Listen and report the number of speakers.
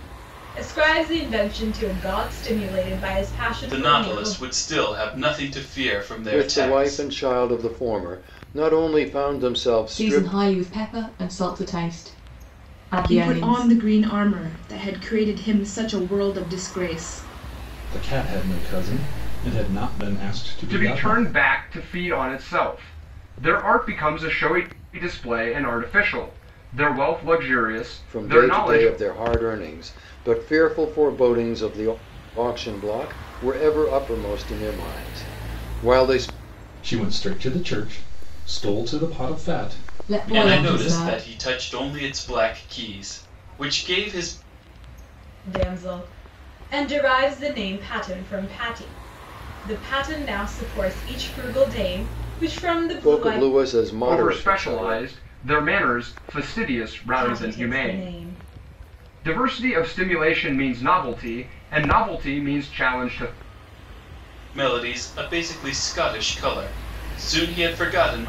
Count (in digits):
7